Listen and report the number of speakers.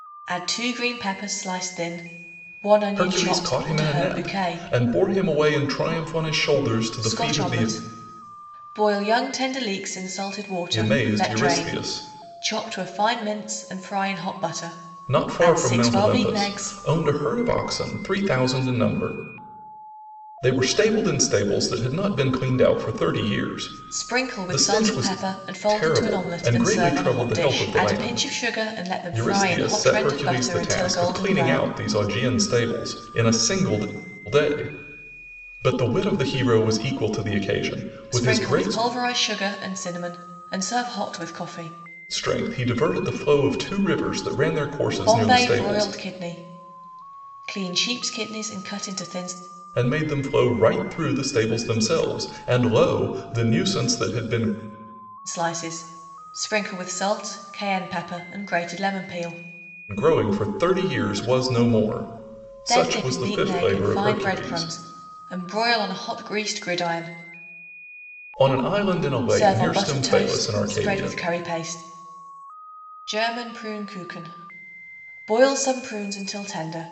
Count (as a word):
two